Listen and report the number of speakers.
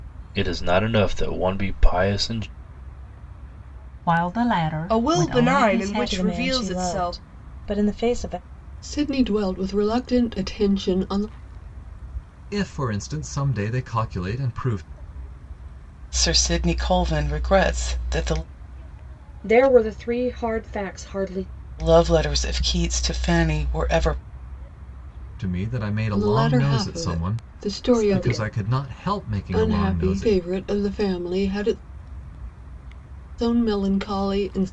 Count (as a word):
eight